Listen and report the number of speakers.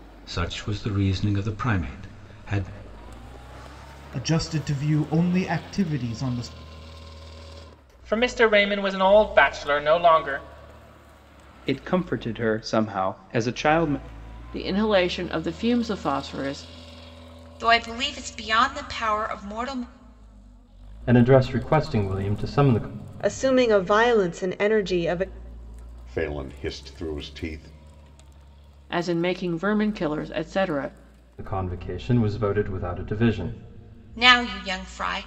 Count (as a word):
nine